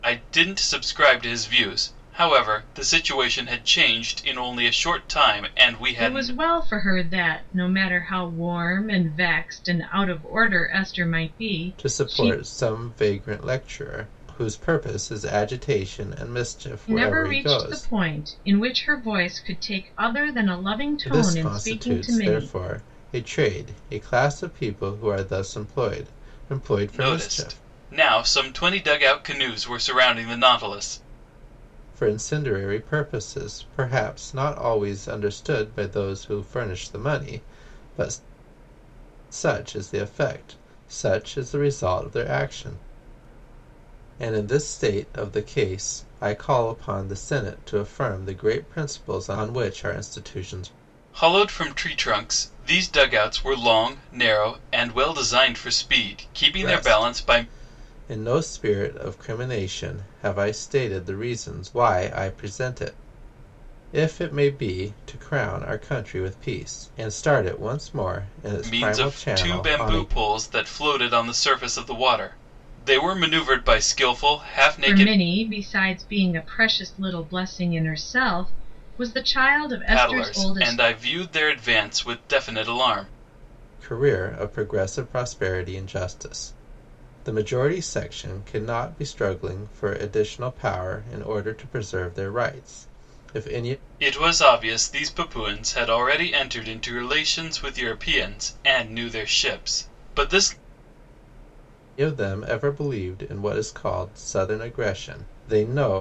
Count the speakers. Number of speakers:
3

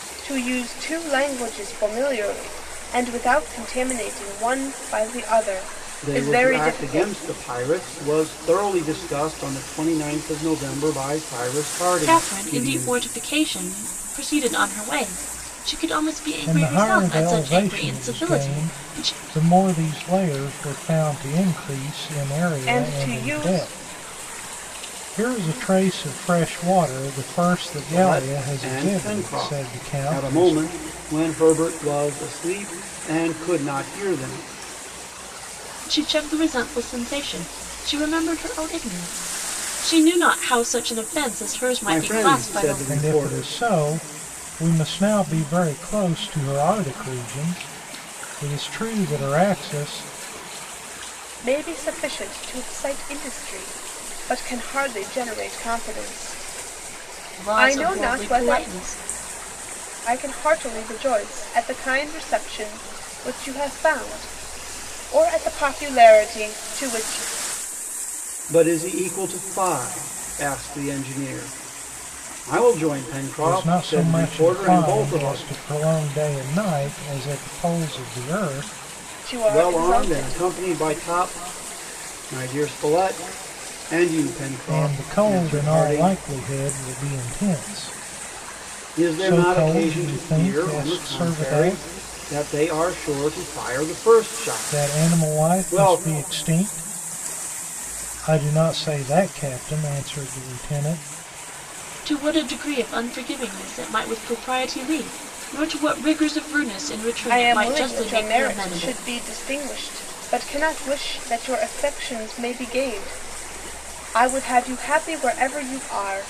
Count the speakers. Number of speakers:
4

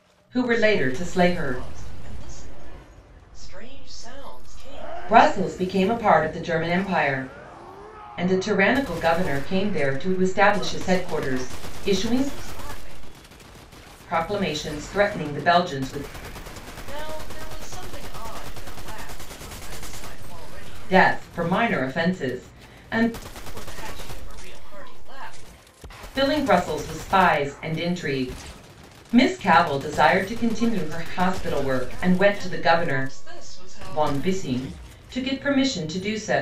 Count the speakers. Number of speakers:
2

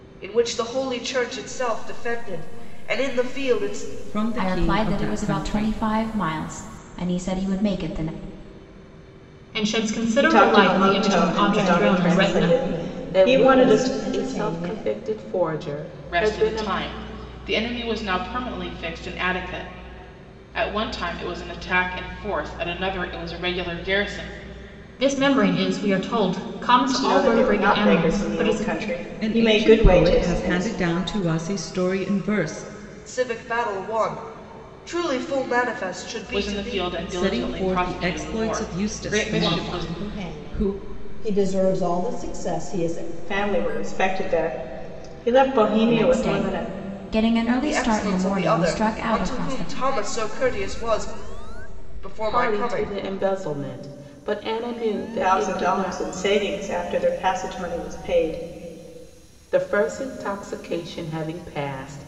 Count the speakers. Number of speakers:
9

